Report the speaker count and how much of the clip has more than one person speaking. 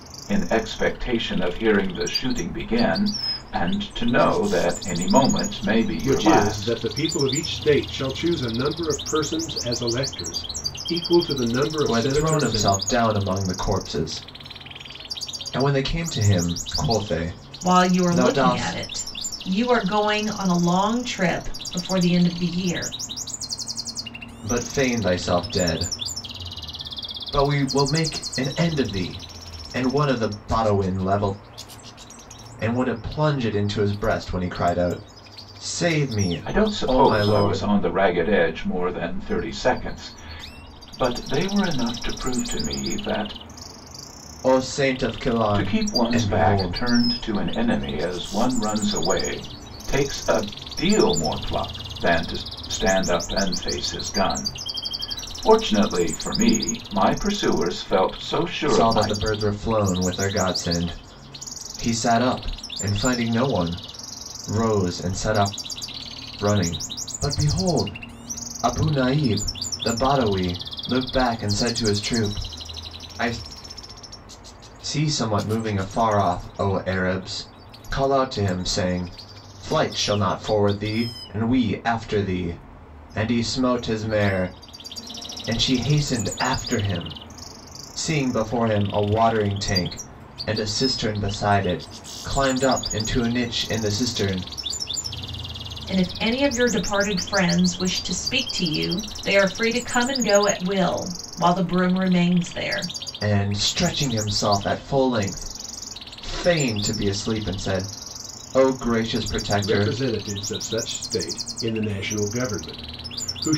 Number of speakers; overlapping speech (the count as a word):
four, about 6%